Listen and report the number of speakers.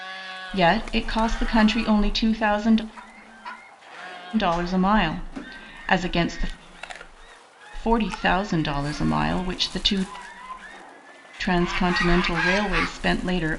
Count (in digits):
1